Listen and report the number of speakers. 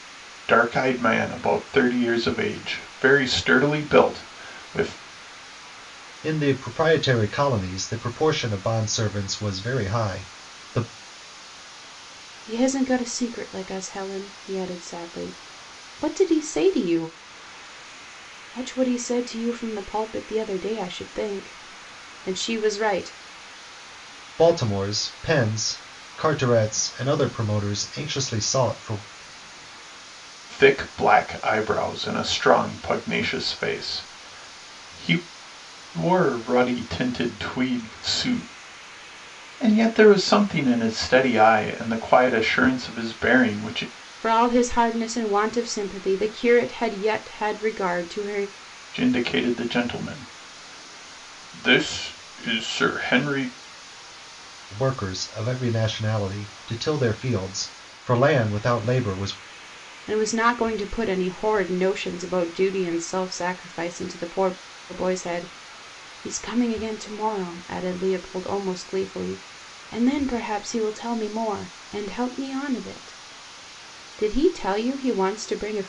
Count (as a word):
three